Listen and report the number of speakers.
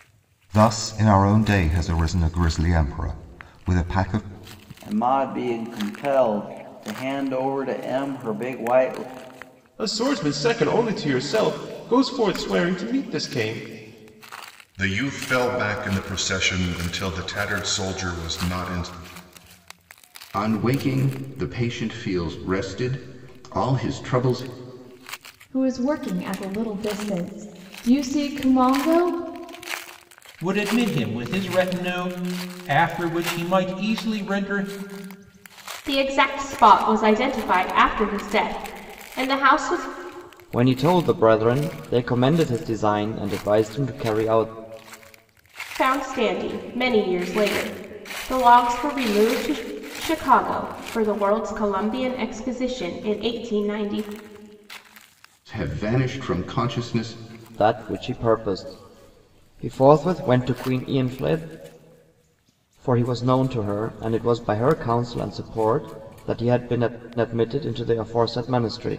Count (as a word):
nine